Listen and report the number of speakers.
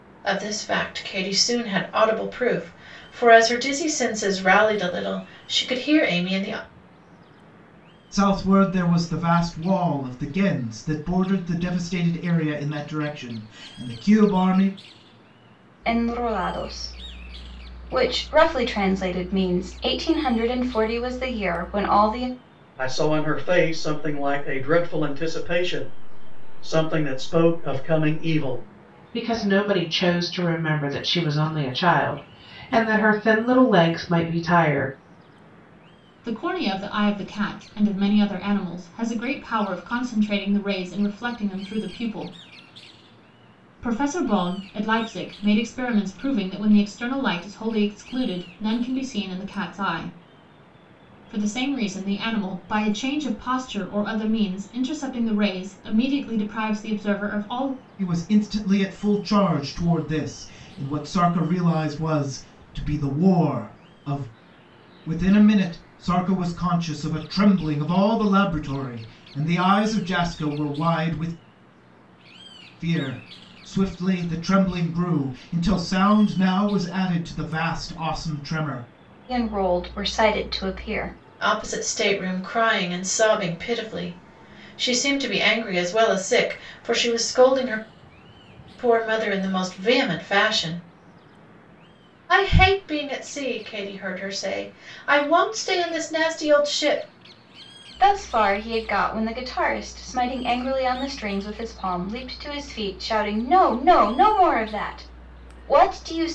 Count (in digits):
6